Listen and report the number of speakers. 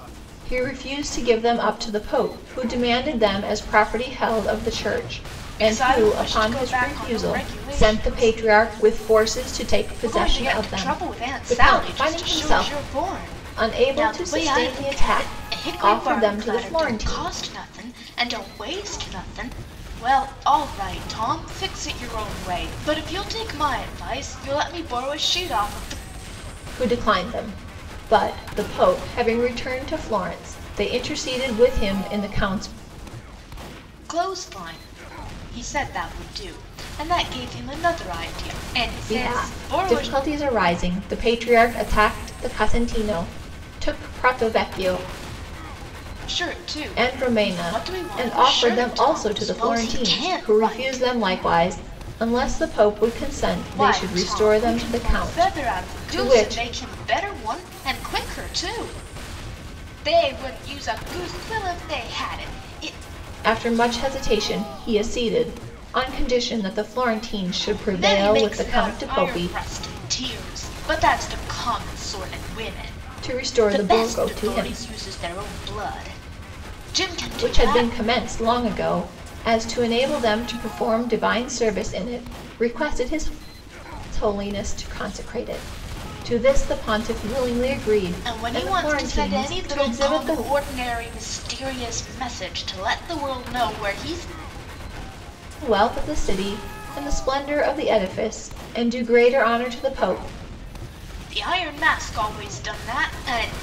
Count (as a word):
two